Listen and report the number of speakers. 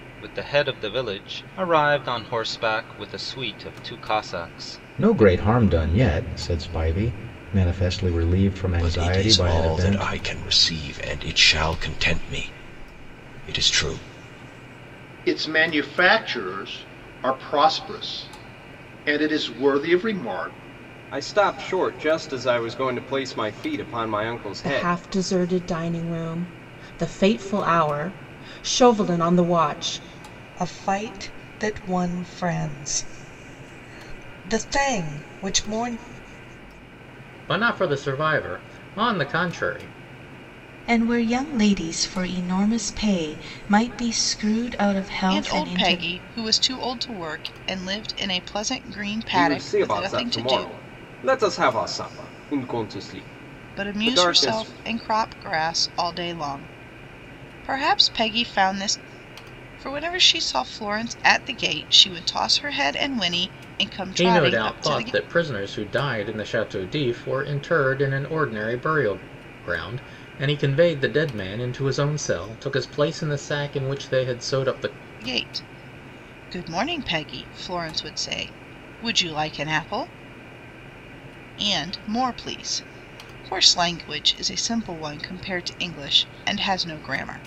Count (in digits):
10